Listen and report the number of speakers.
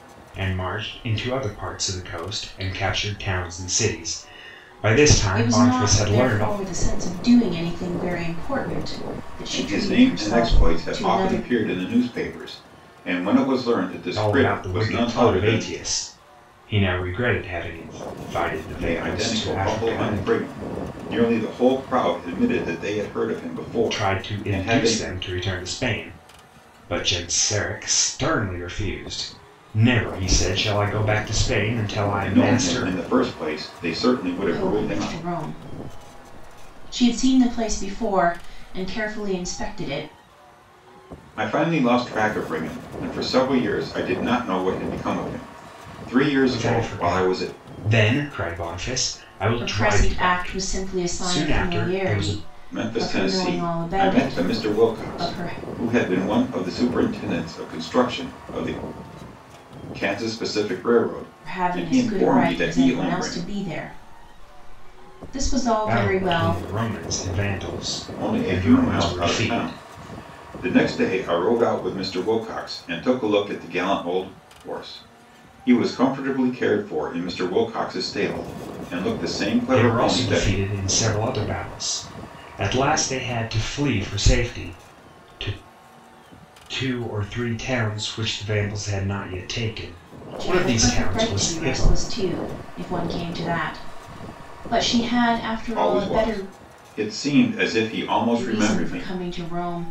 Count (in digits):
3